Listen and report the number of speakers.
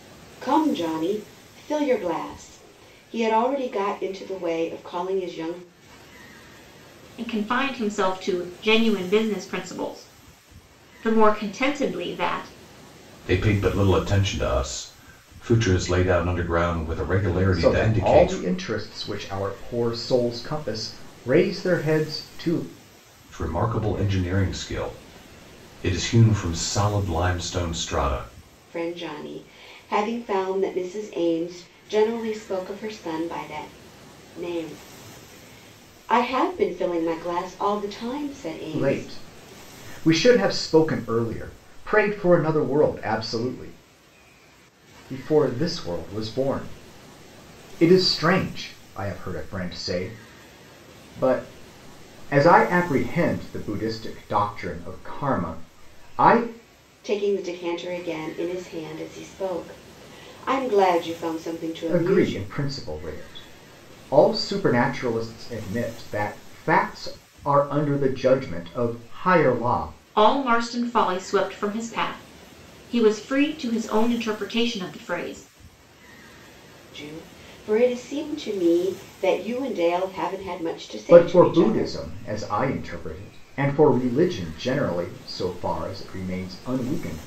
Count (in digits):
4